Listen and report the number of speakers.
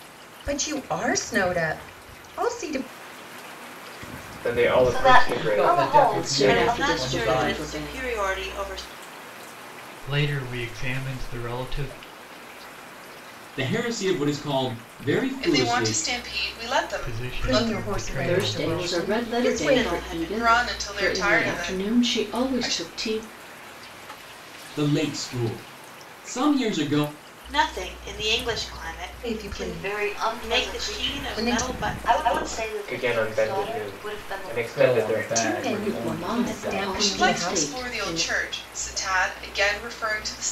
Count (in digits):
9